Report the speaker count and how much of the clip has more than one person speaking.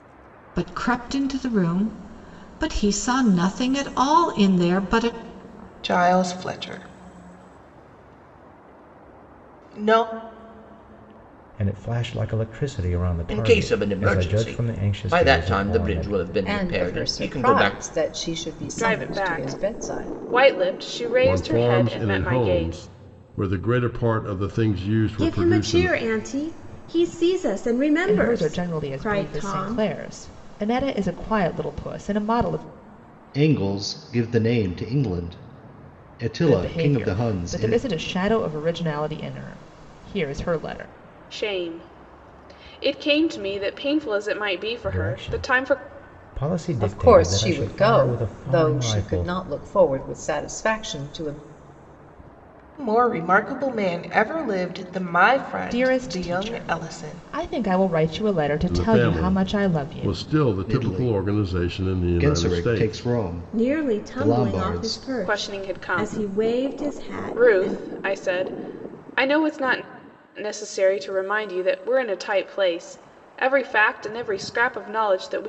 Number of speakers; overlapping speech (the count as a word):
ten, about 33%